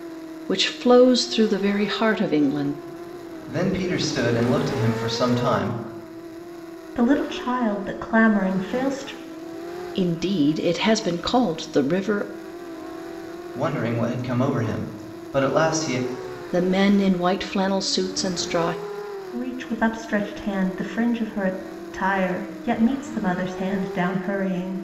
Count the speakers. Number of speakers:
3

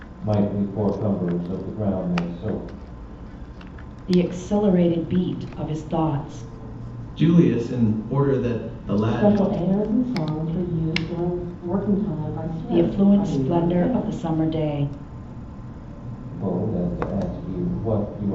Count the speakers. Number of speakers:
4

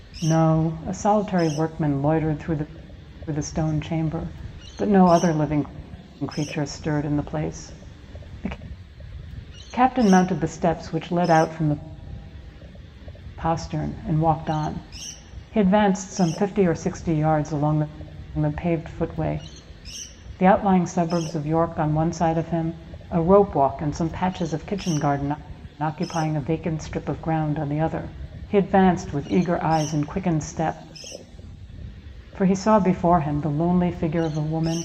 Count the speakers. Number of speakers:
1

